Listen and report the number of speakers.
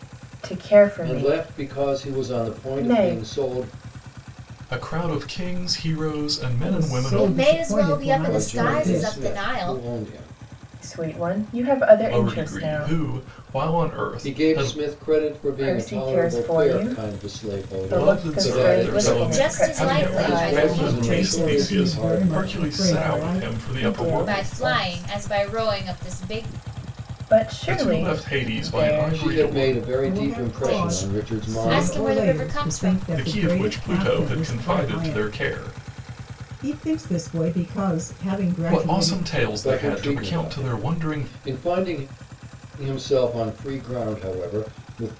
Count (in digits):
5